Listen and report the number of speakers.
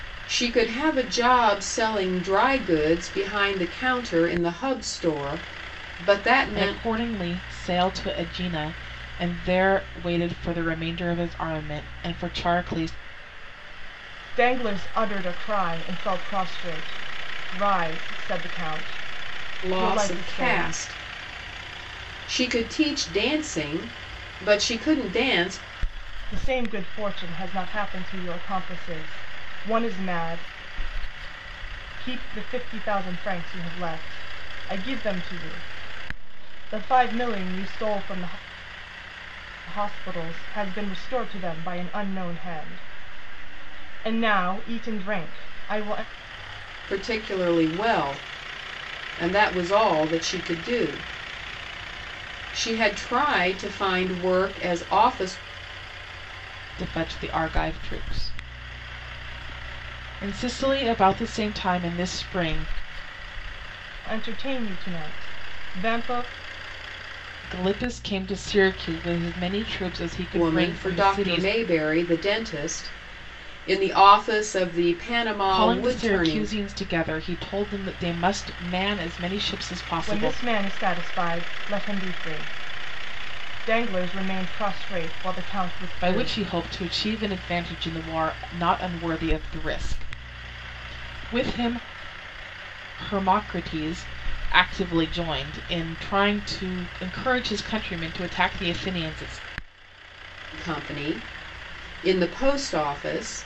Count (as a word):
three